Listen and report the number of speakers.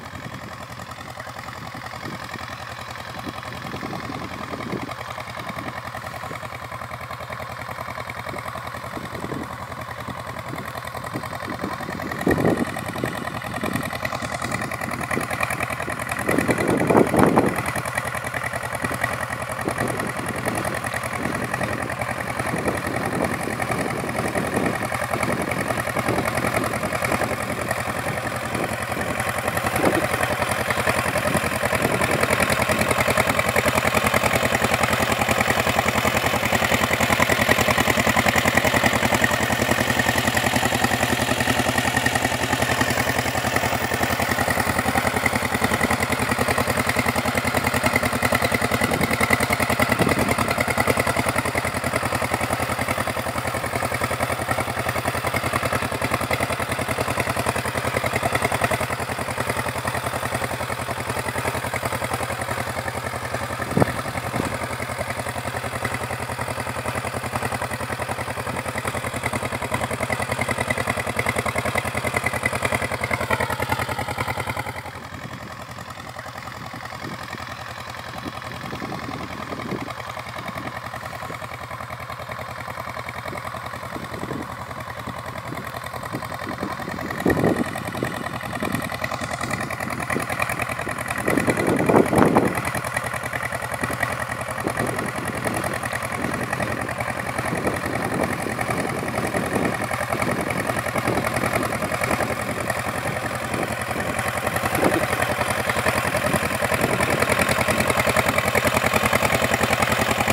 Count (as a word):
zero